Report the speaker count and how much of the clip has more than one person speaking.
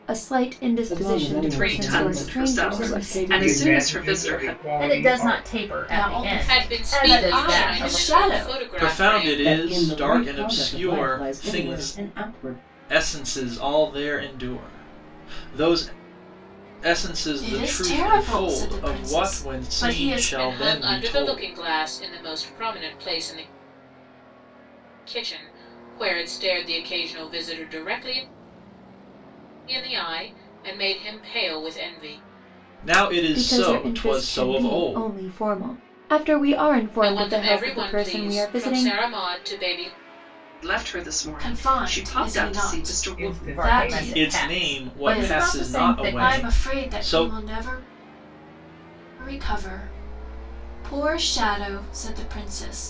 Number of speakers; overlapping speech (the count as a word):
nine, about 46%